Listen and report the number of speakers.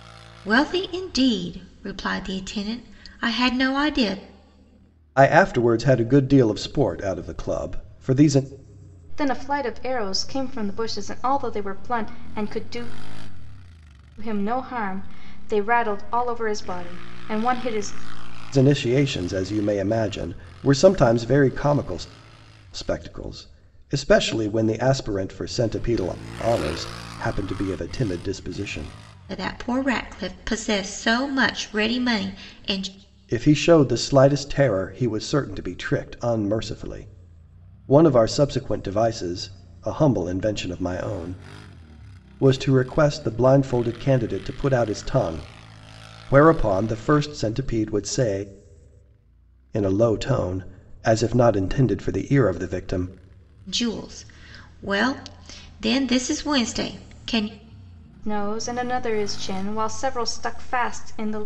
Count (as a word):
three